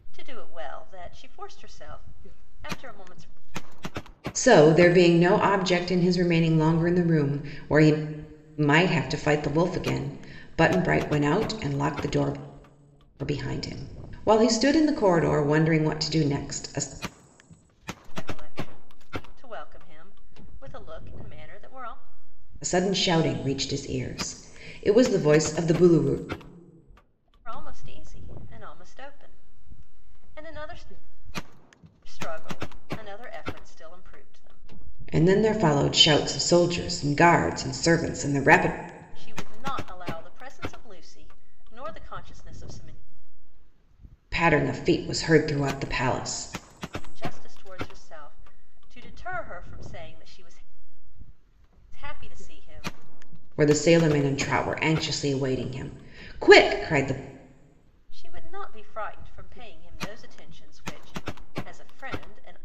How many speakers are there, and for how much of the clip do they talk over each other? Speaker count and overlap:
2, no overlap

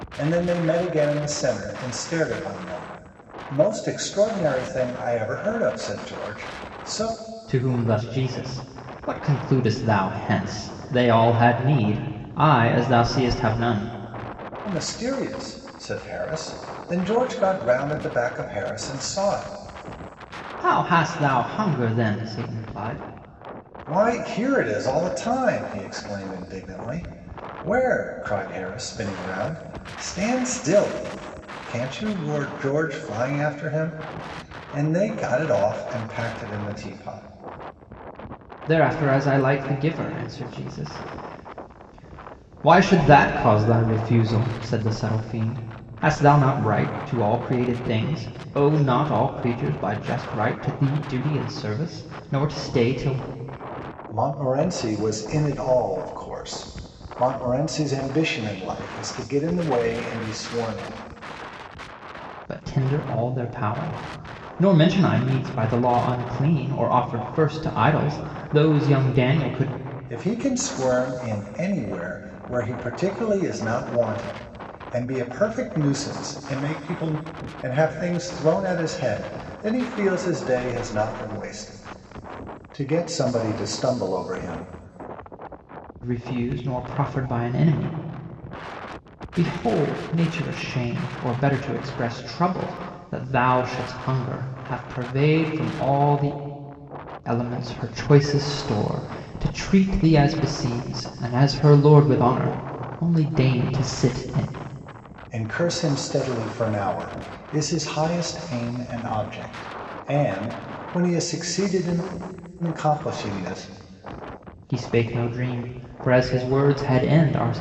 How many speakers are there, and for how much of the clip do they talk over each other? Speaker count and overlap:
2, no overlap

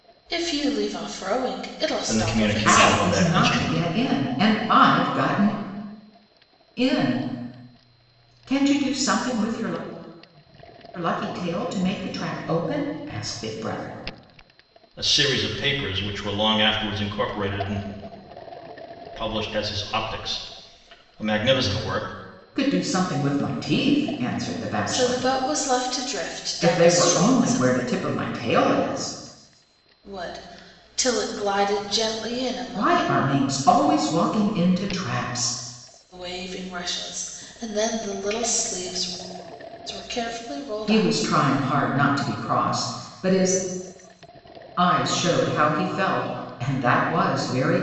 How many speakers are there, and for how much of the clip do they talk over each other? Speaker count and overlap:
3, about 9%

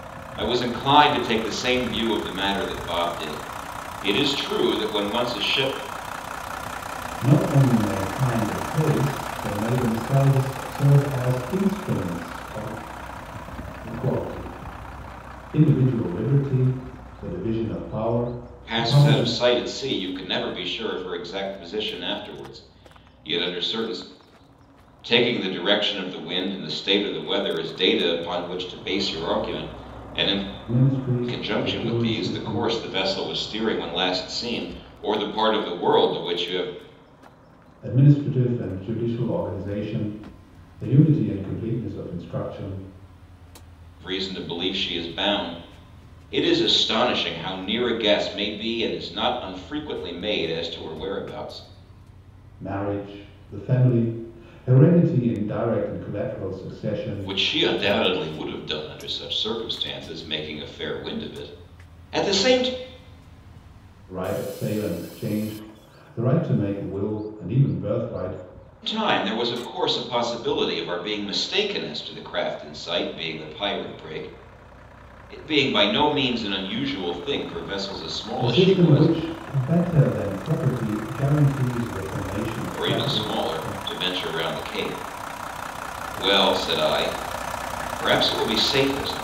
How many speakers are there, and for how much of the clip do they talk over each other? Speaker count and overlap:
2, about 6%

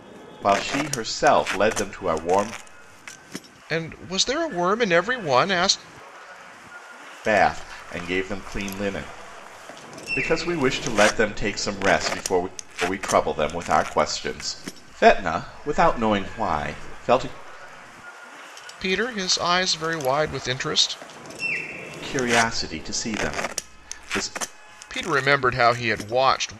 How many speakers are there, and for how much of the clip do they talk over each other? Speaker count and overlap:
2, no overlap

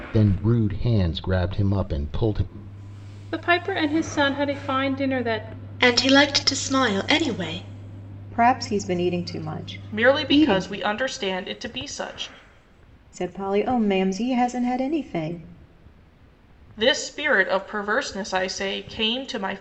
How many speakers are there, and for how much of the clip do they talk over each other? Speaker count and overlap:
5, about 4%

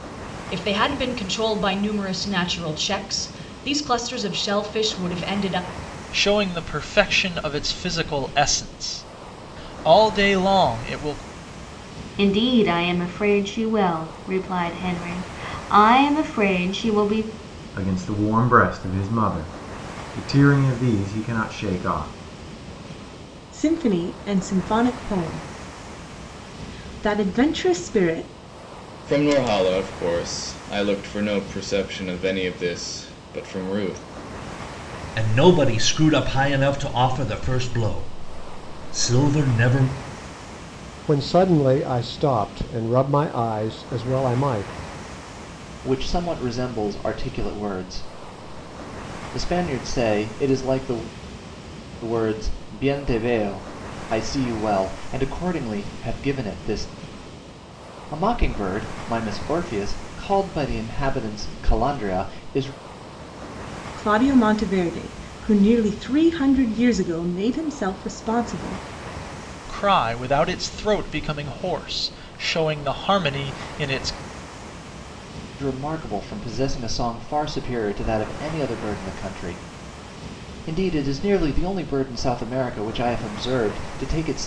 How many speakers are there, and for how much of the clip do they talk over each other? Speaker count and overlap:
9, no overlap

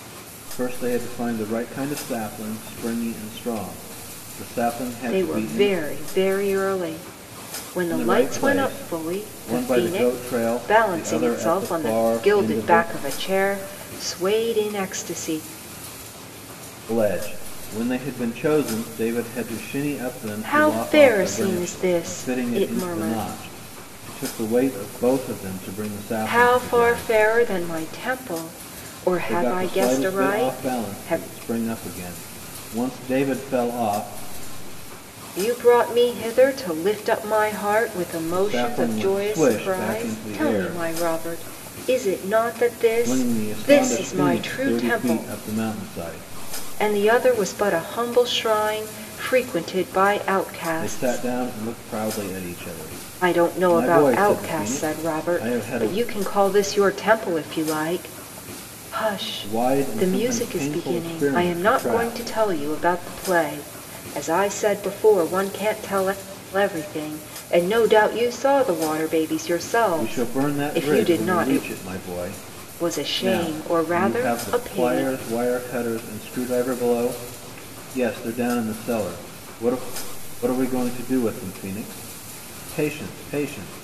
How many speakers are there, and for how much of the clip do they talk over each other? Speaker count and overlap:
2, about 32%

